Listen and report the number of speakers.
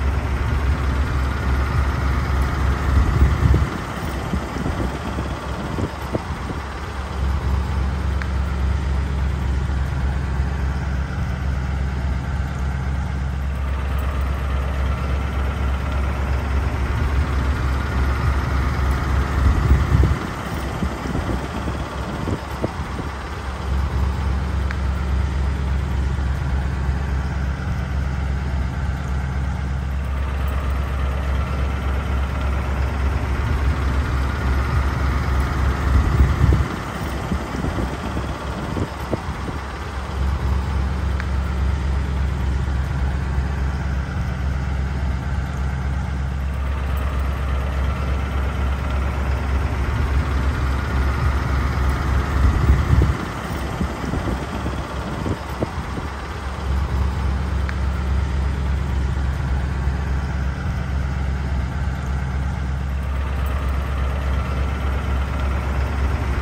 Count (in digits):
0